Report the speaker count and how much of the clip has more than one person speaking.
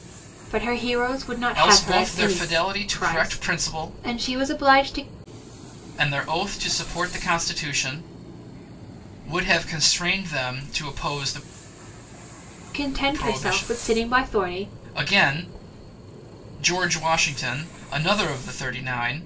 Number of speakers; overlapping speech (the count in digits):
2, about 19%